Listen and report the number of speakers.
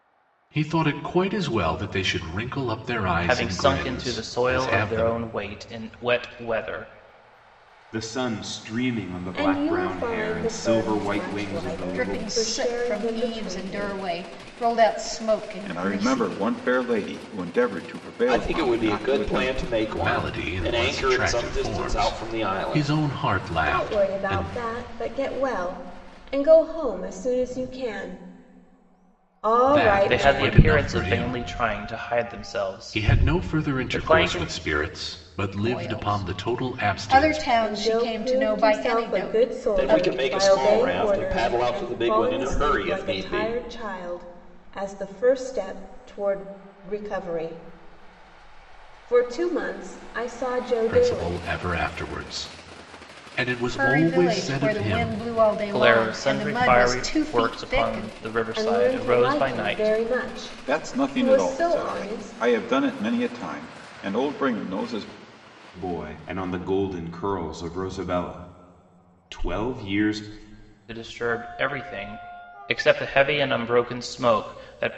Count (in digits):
7